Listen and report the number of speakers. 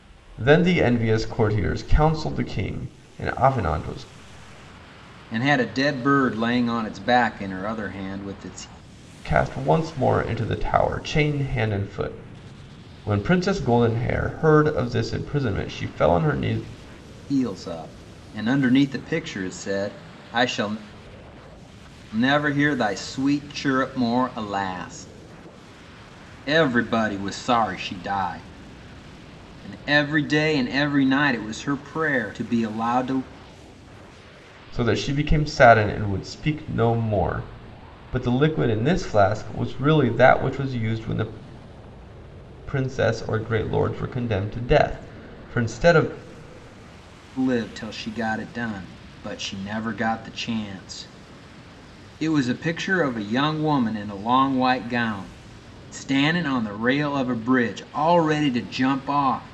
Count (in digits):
2